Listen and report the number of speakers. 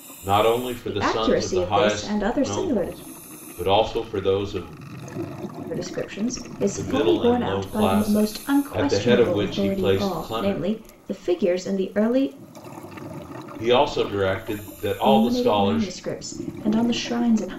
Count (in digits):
2